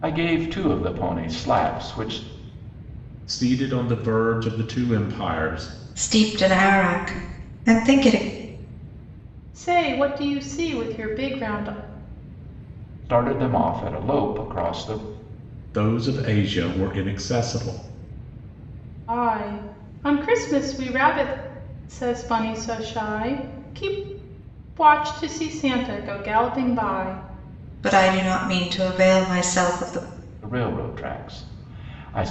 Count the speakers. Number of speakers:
4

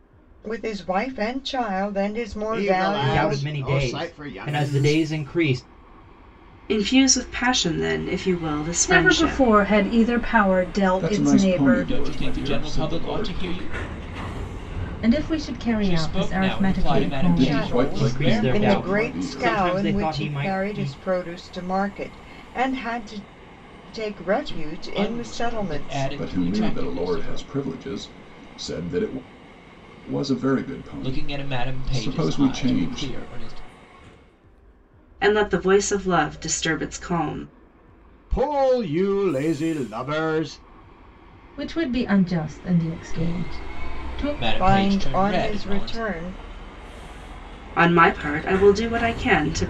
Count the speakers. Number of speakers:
8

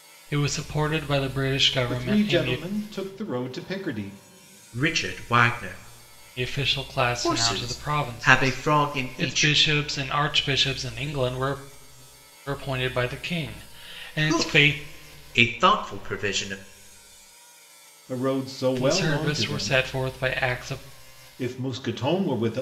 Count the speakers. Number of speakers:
3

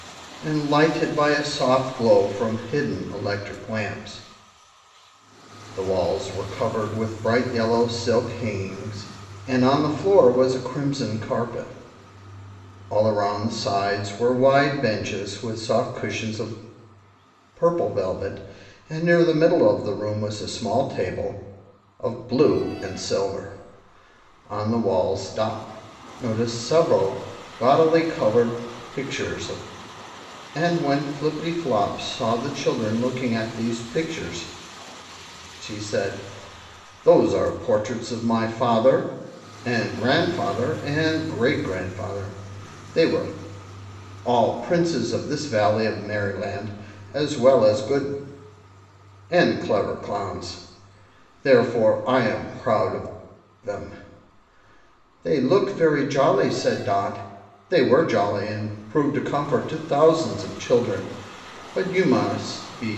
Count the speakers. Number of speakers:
1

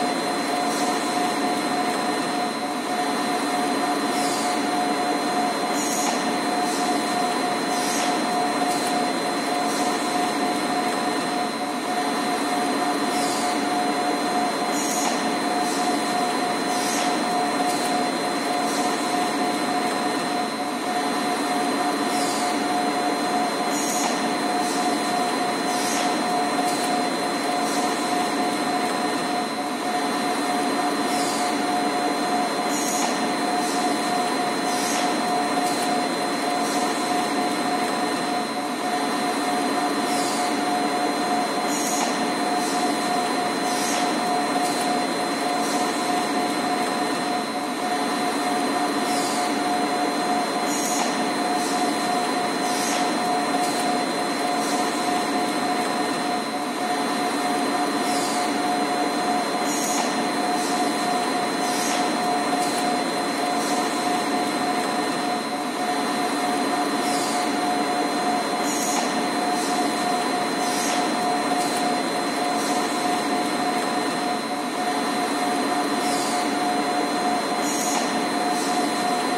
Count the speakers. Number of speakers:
0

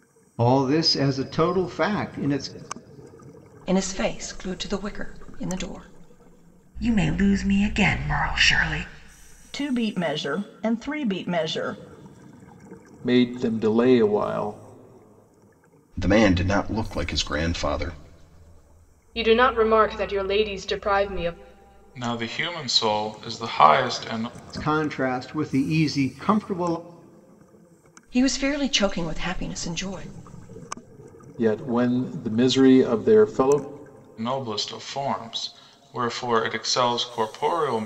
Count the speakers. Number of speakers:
8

